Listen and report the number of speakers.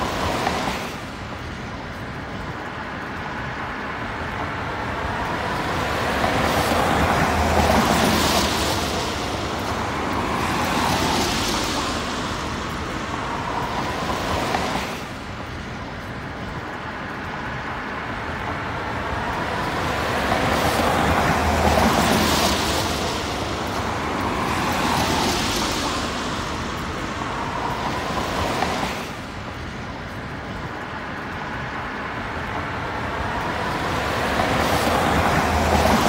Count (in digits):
0